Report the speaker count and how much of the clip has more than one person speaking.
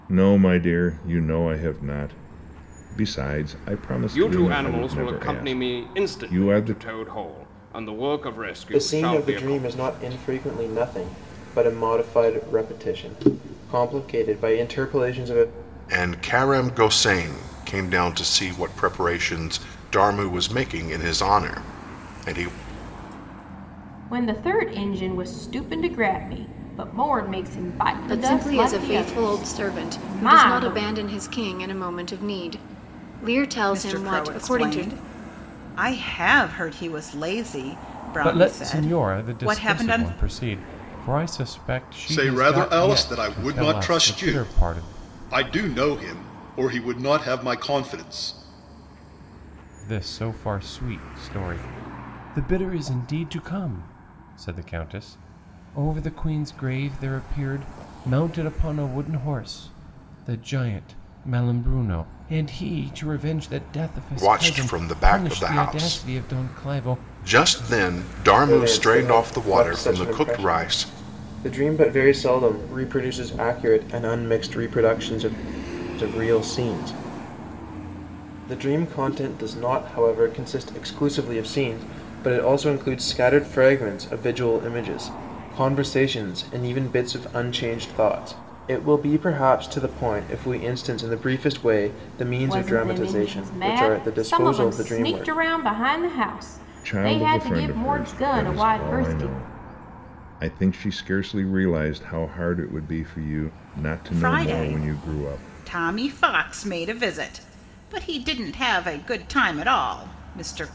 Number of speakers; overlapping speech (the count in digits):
9, about 23%